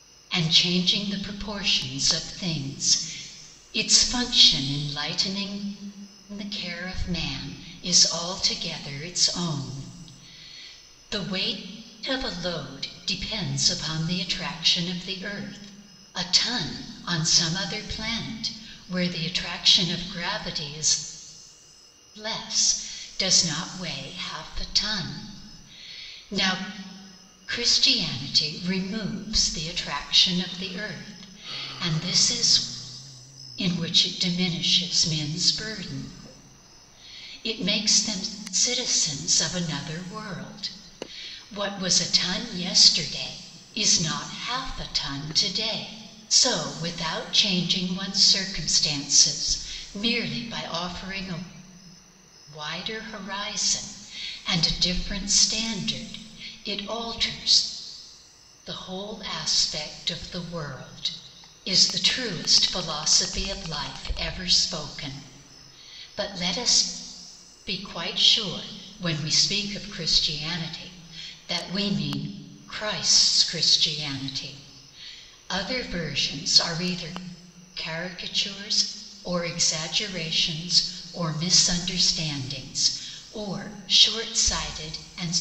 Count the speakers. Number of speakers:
one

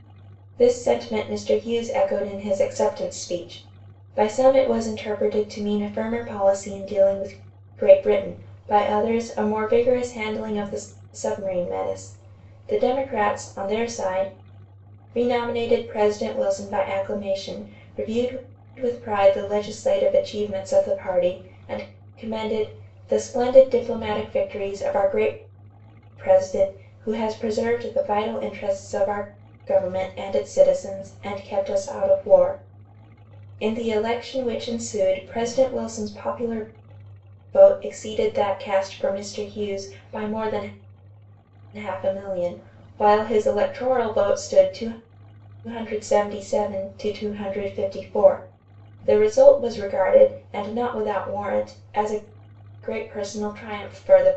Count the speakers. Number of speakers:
one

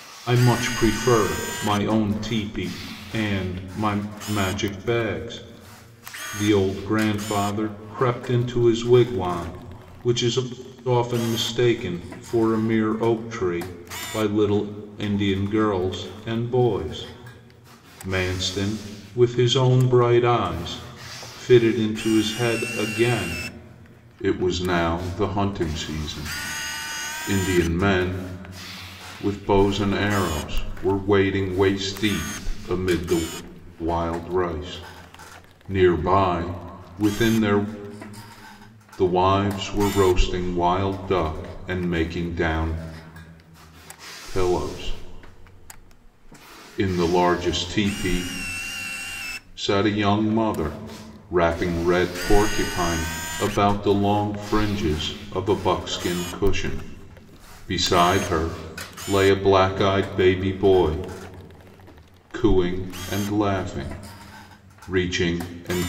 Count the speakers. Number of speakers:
one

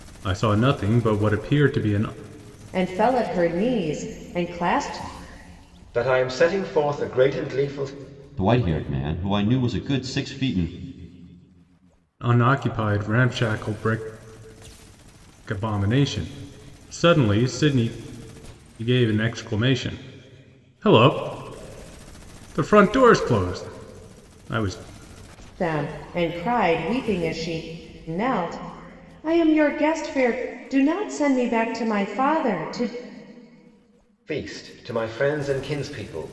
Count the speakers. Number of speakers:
four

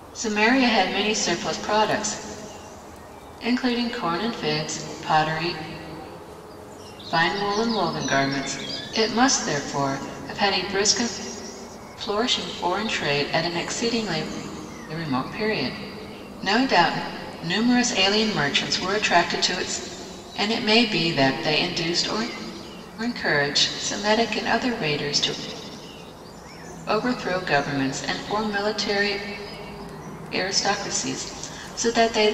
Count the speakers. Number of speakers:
one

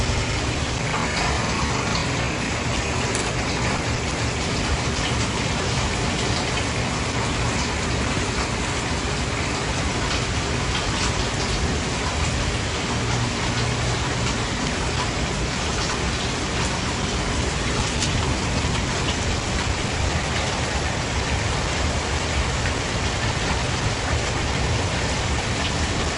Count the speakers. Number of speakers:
zero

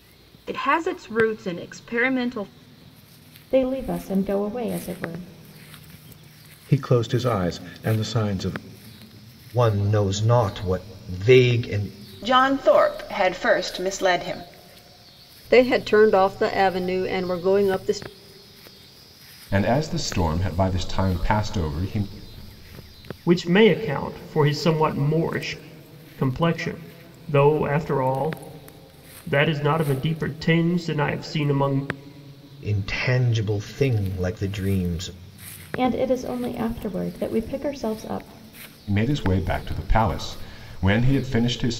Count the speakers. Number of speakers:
eight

